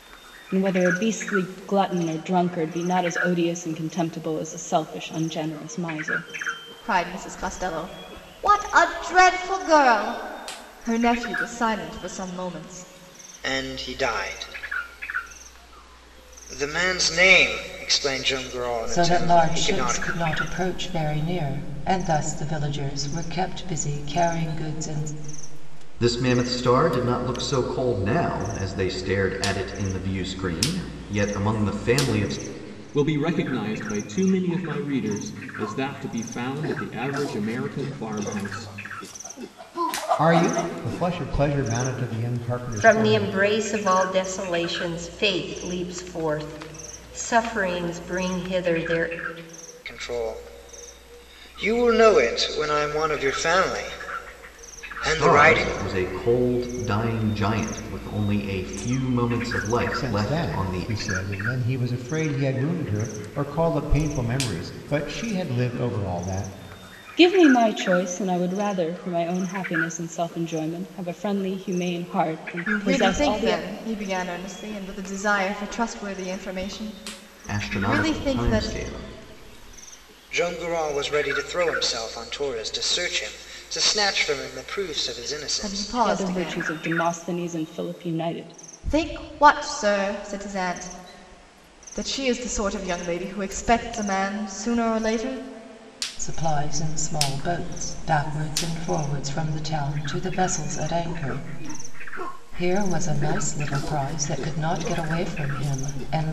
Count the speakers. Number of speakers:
8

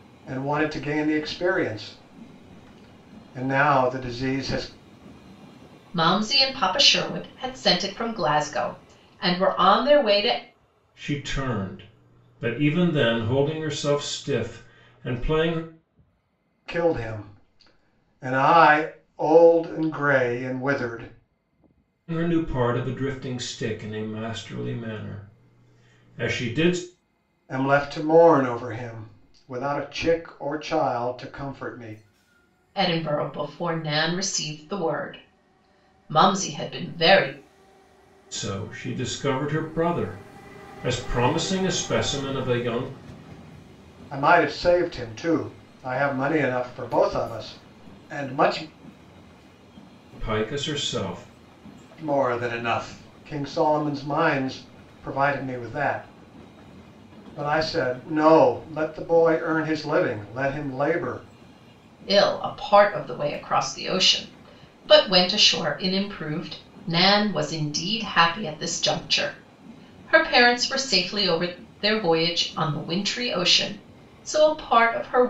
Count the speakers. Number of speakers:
3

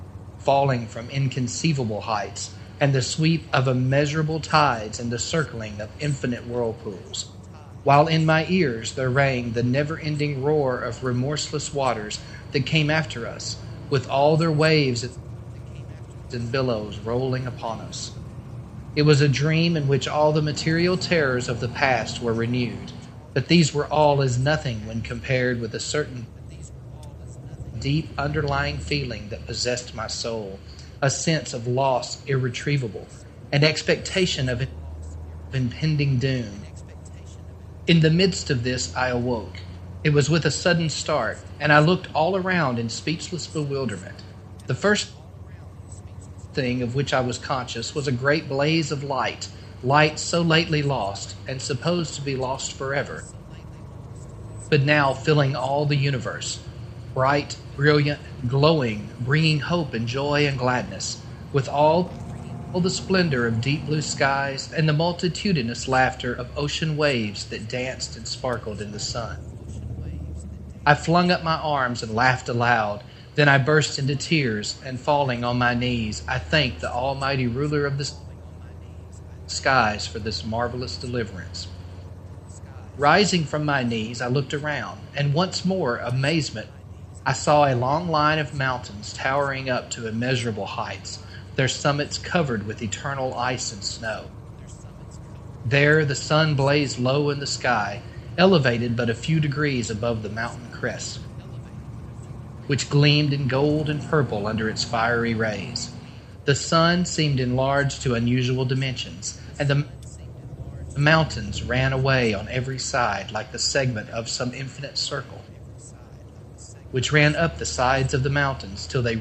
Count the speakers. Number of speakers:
1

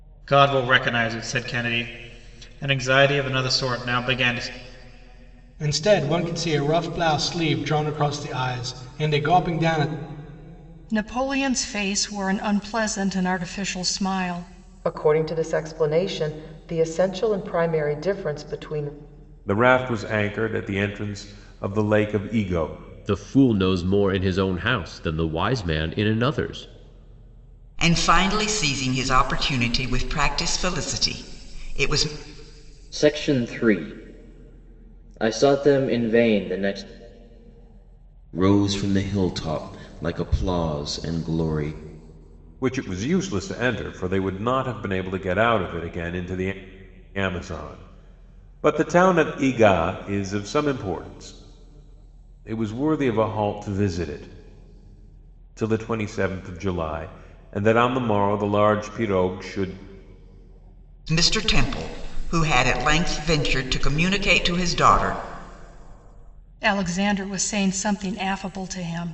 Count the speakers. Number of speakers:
9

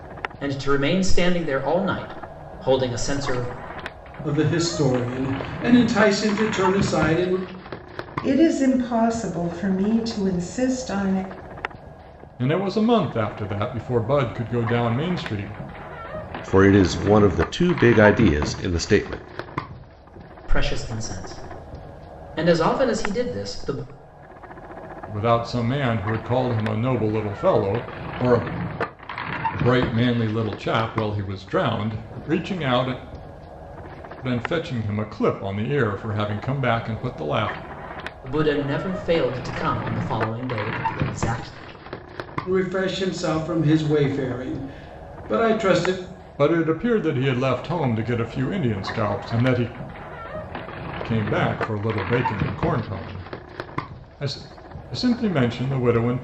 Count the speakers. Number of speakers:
5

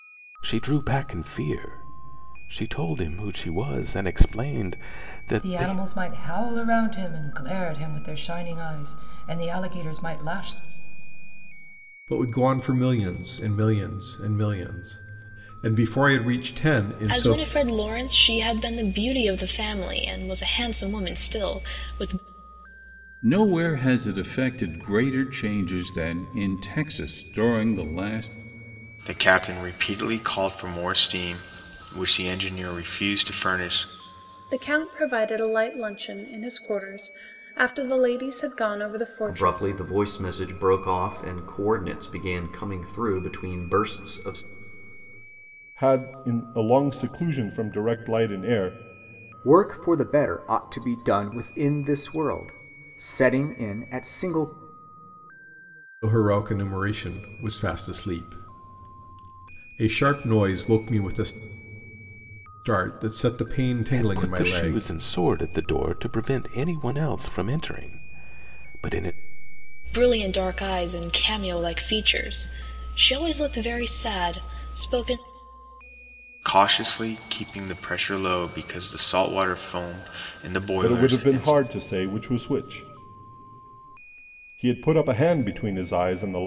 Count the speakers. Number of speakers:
10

